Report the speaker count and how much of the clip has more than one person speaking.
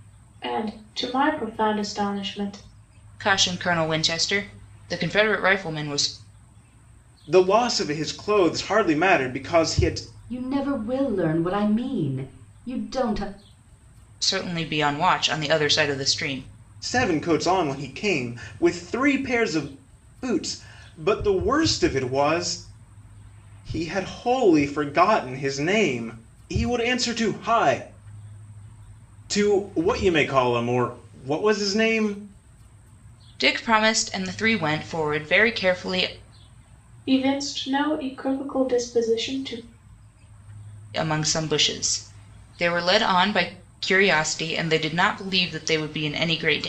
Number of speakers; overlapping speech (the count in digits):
4, no overlap